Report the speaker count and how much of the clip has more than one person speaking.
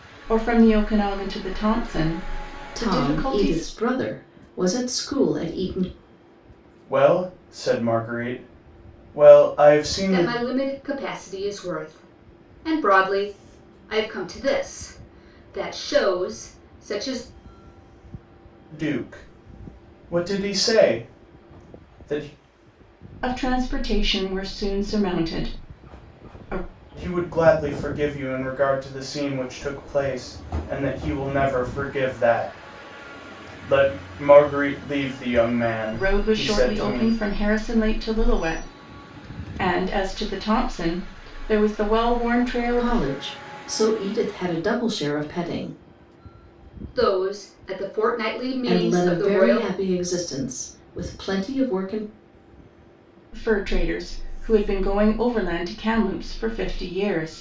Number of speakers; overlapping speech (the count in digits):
4, about 7%